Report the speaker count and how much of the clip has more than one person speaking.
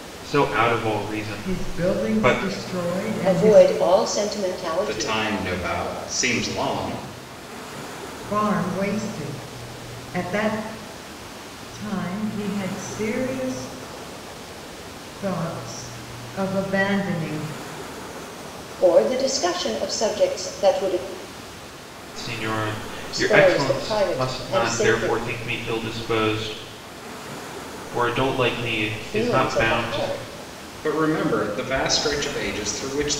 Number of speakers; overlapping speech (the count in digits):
4, about 16%